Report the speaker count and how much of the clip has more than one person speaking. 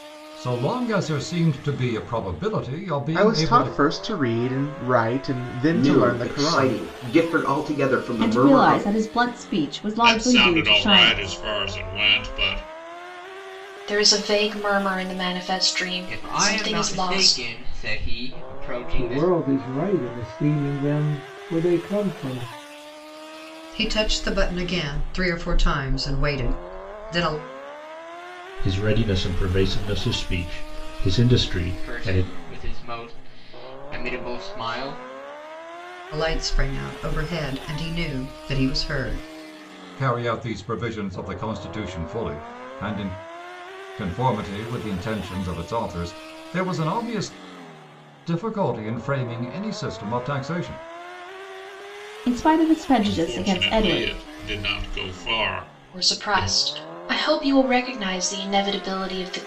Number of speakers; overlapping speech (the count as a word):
ten, about 14%